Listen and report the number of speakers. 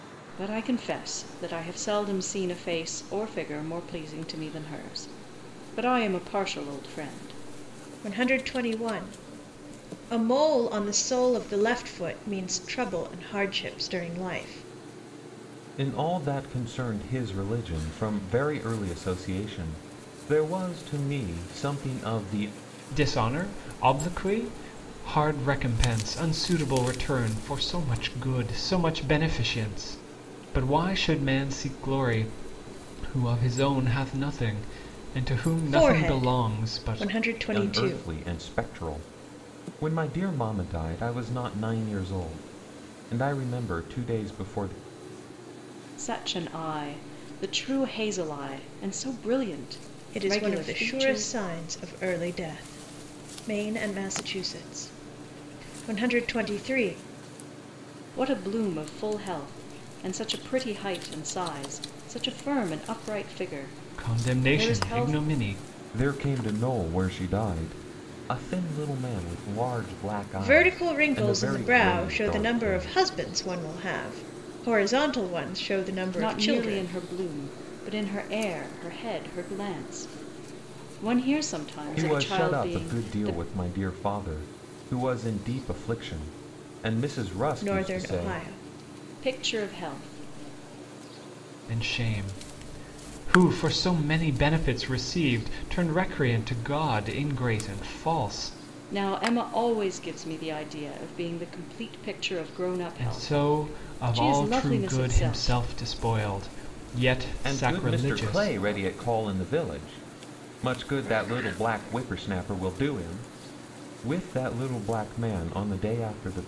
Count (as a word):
four